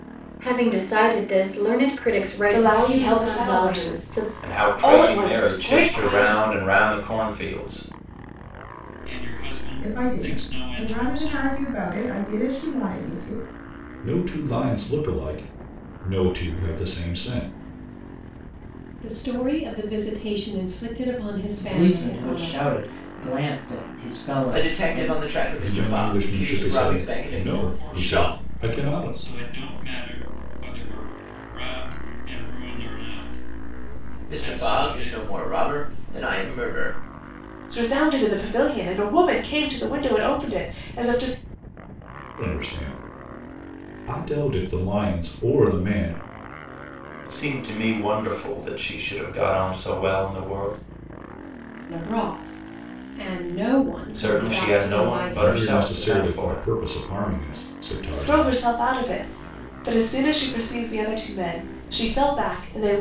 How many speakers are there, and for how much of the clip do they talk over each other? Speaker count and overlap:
9, about 24%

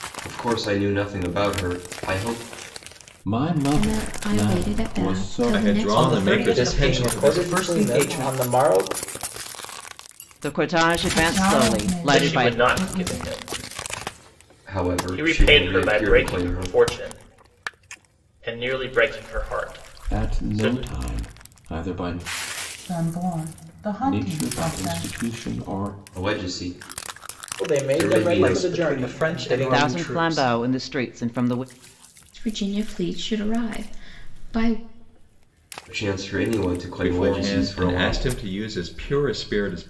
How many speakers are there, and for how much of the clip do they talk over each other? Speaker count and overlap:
9, about 36%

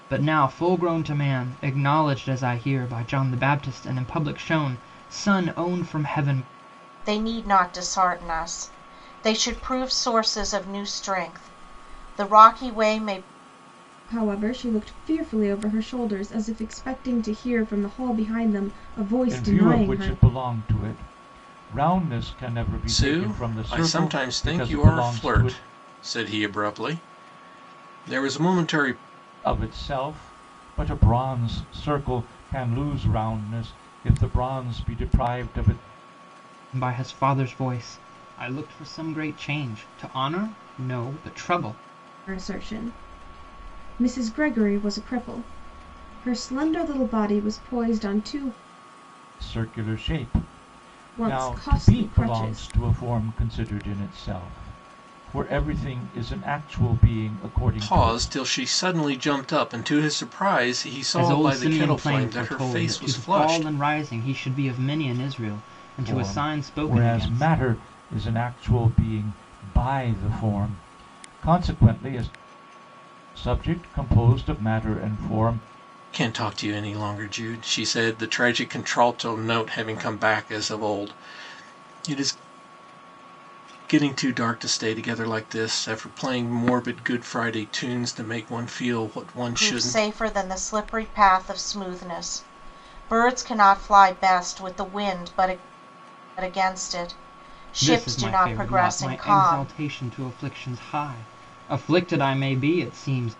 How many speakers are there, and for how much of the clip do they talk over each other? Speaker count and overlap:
5, about 12%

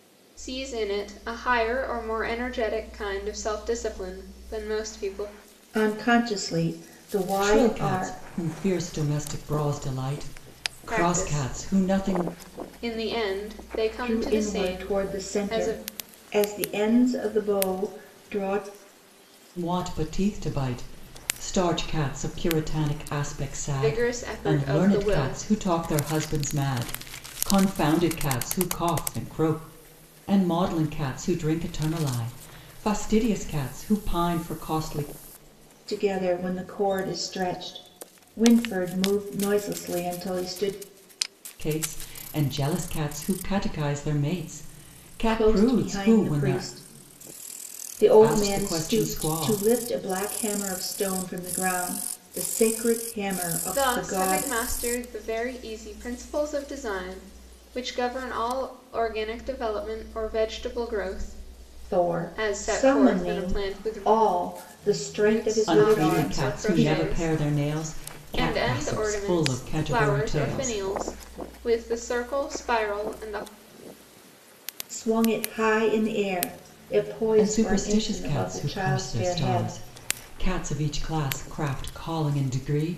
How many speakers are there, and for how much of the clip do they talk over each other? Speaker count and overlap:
3, about 23%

